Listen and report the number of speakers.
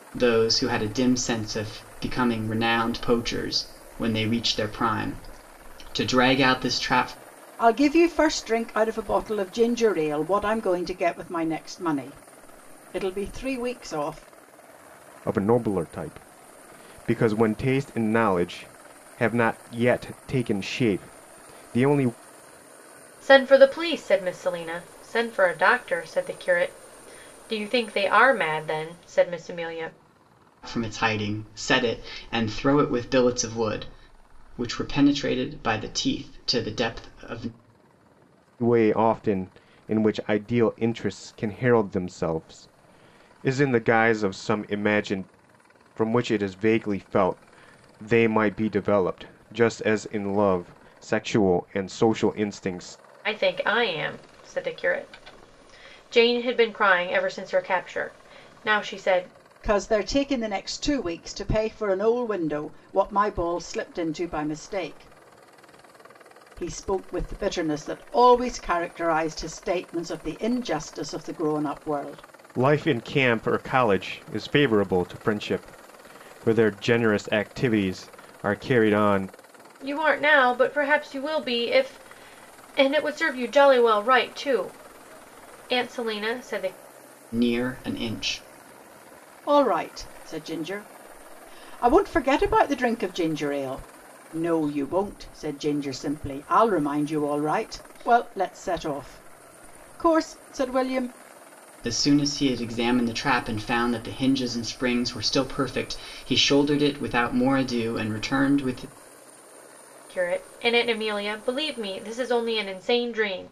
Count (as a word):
four